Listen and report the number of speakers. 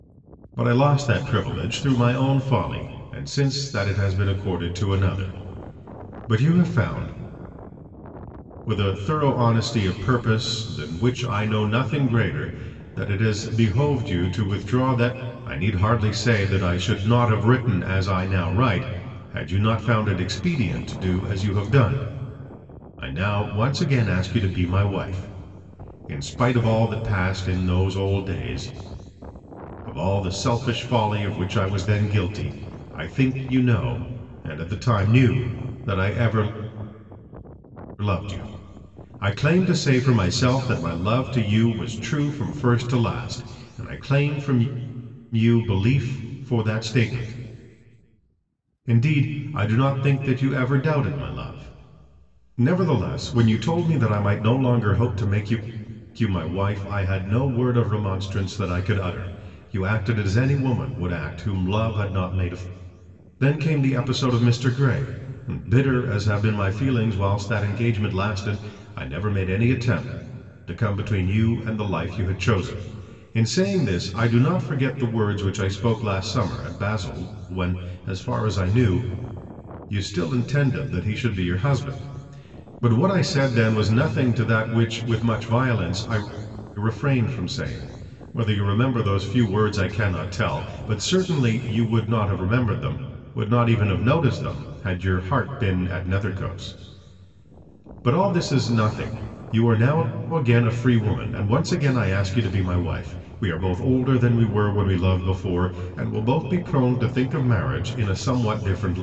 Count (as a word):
one